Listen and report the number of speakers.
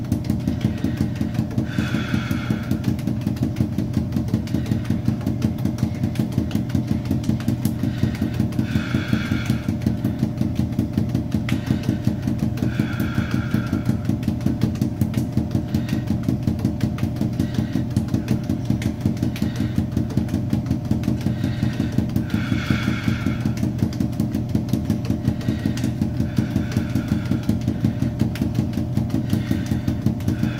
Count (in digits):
0